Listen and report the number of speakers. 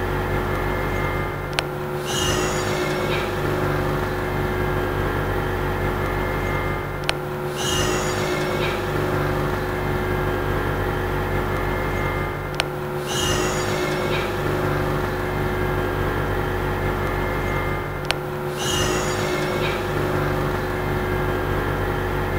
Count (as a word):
zero